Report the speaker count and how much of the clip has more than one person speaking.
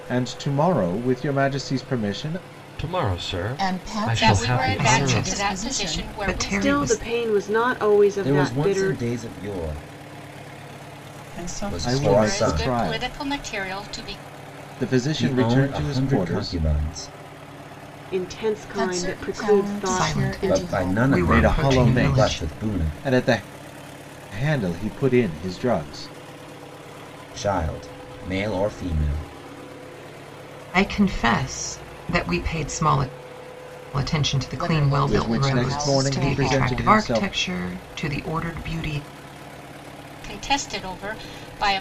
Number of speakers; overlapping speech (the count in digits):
8, about 34%